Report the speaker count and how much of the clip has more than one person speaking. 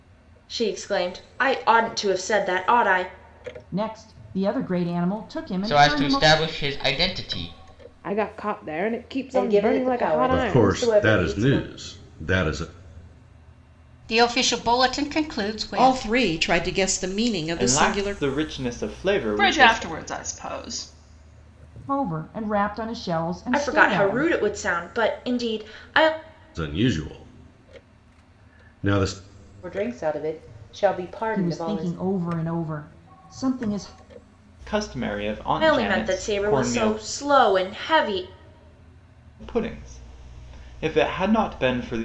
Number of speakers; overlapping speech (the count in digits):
10, about 18%